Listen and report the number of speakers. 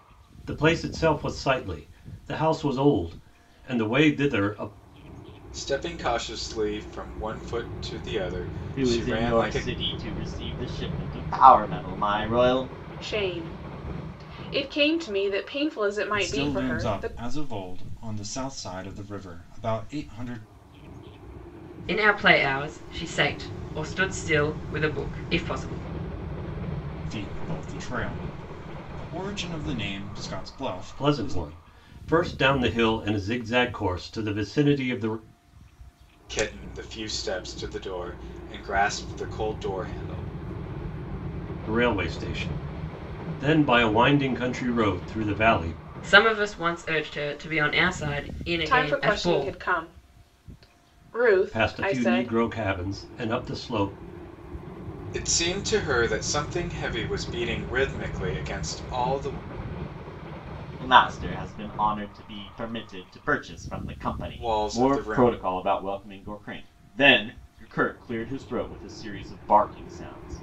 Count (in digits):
6